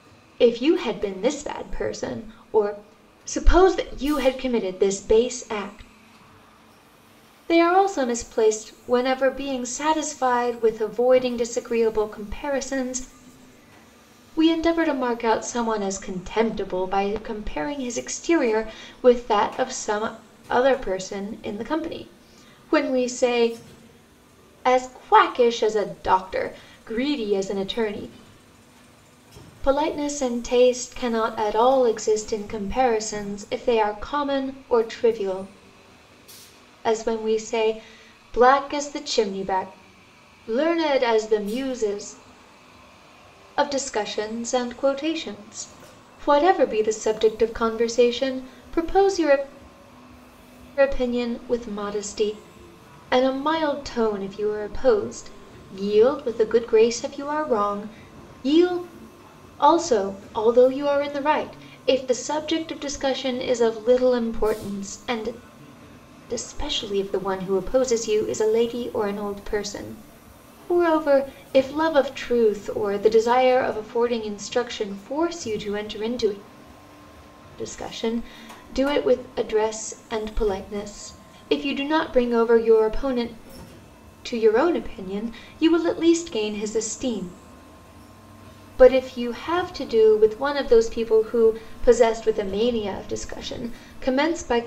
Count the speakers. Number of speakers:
one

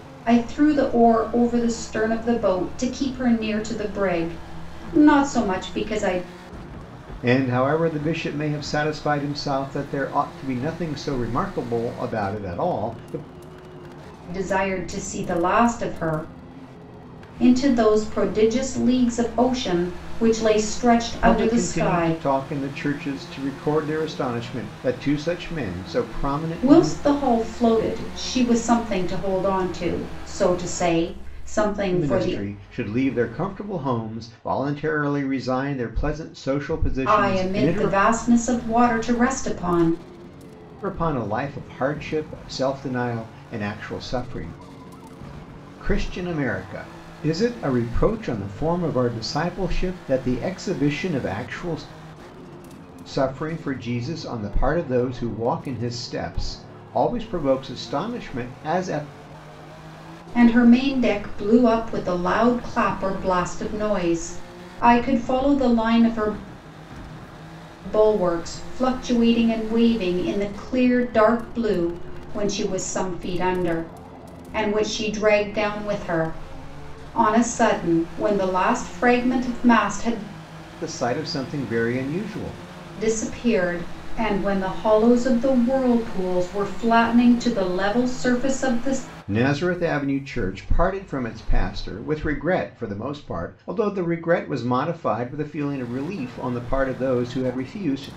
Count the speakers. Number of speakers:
two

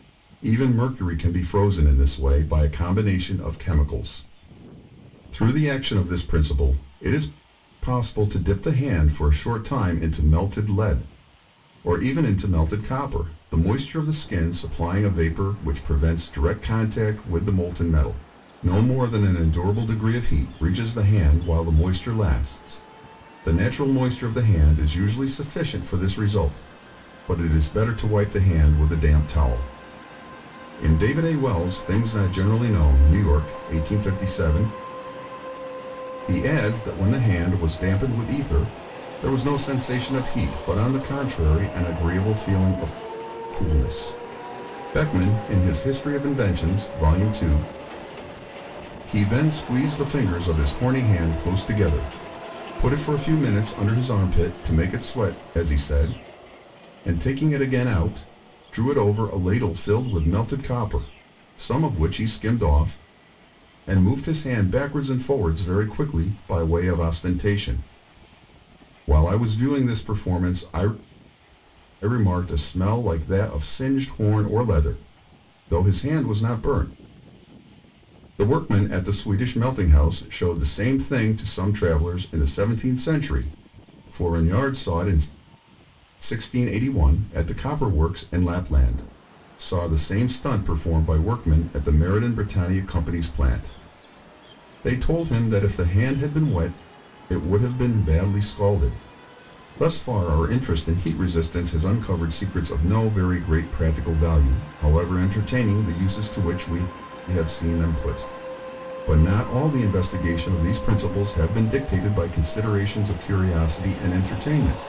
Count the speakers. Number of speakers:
one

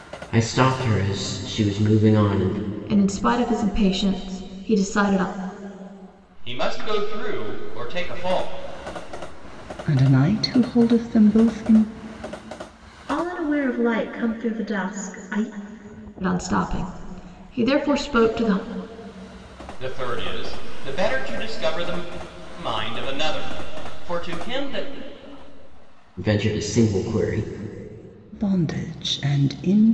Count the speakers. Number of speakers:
five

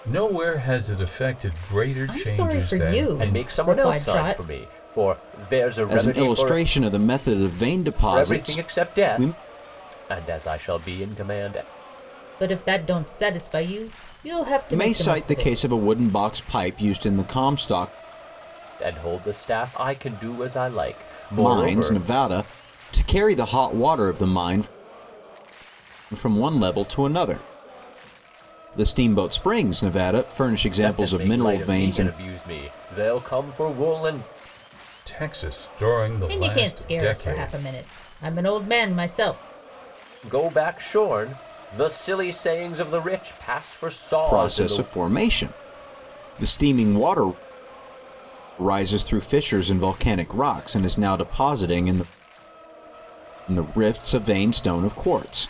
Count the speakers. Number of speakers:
four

